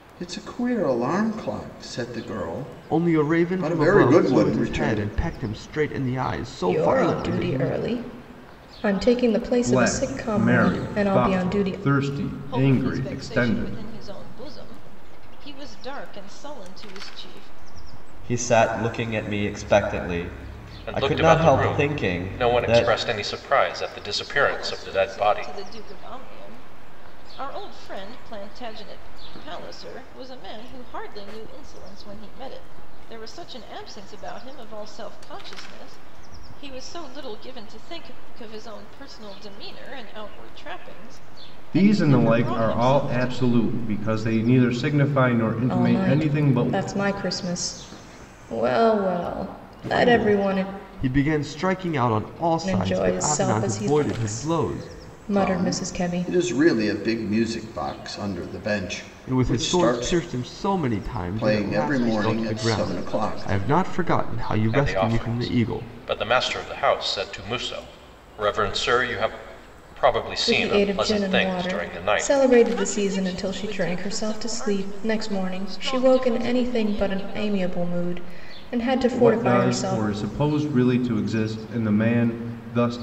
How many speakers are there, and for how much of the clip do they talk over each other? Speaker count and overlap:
7, about 36%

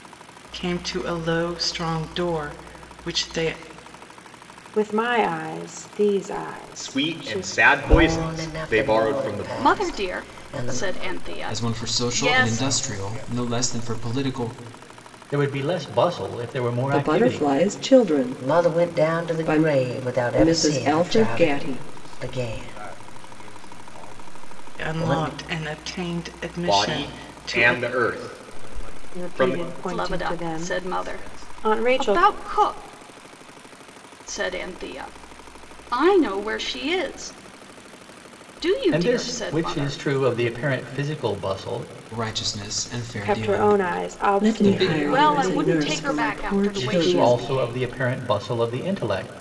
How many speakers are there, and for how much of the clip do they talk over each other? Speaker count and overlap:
9, about 47%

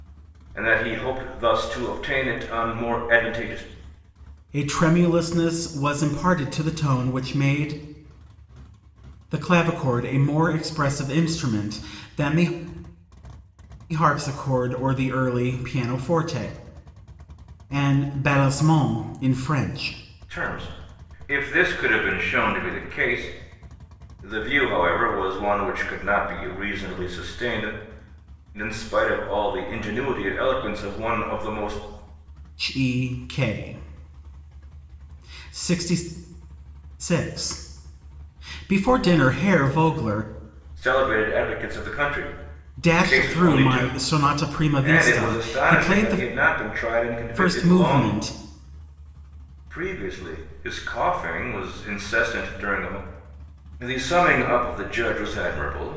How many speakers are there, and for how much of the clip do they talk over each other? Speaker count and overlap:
2, about 6%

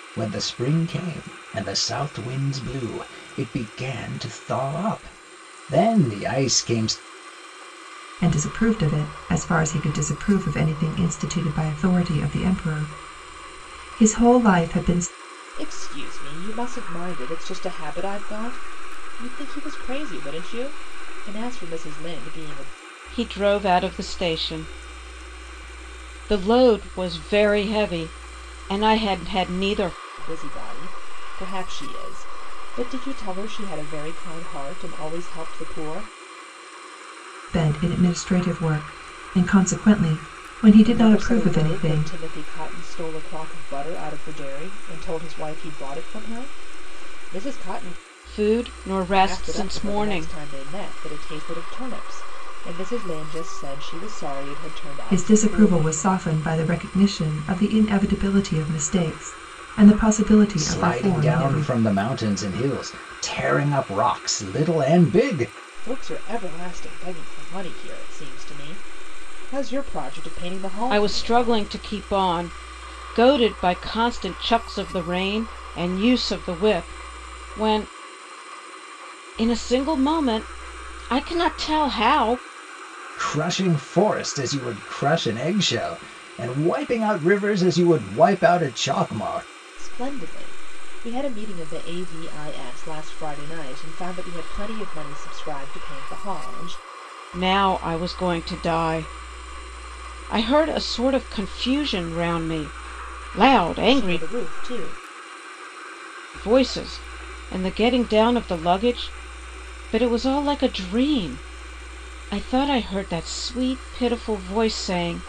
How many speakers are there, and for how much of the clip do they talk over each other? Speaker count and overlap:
4, about 5%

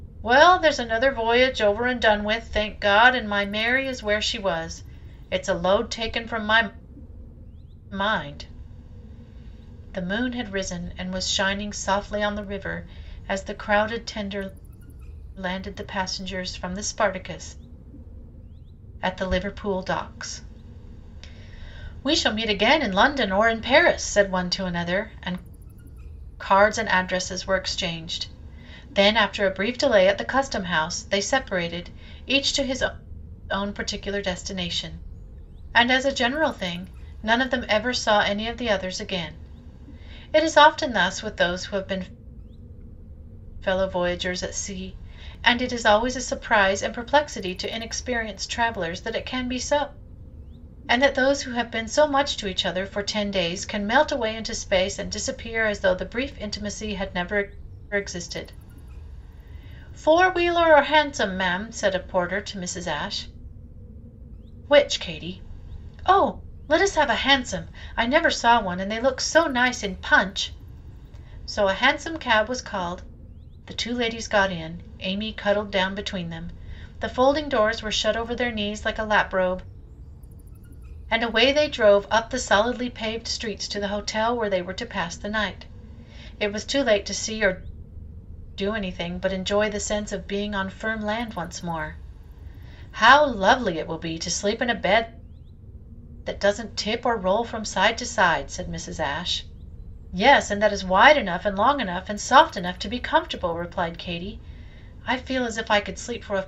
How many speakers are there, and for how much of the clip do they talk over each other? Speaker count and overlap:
1, no overlap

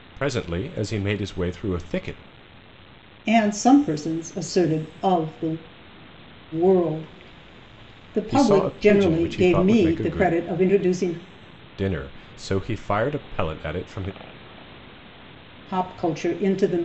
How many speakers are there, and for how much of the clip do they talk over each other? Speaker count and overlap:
2, about 13%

